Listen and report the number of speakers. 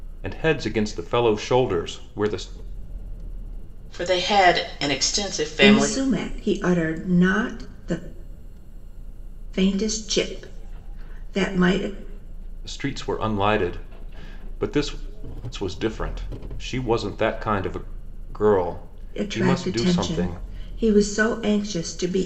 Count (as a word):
three